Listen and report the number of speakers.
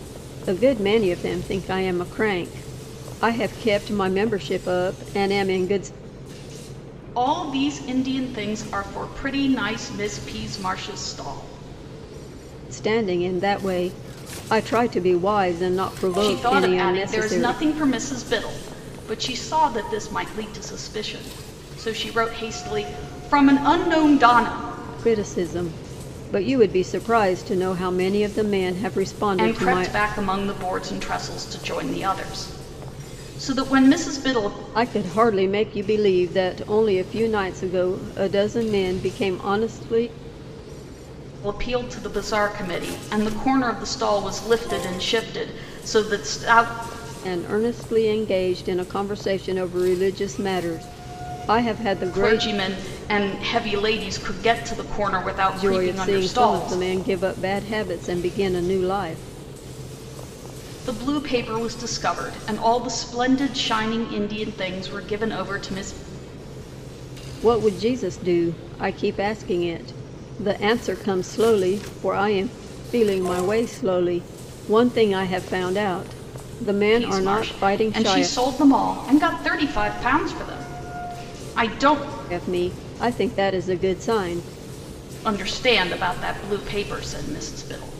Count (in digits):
2